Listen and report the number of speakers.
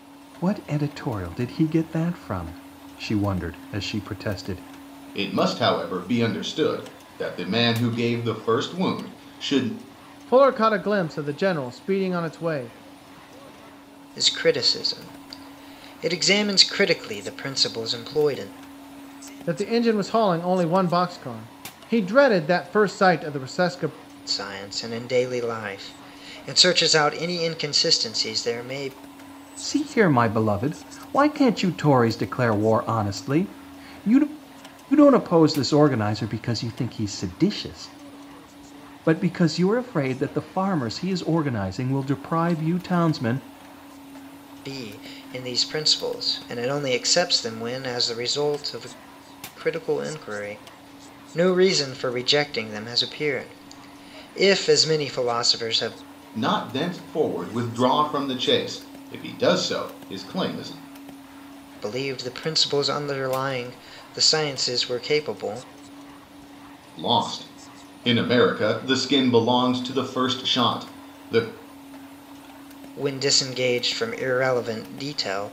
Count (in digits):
4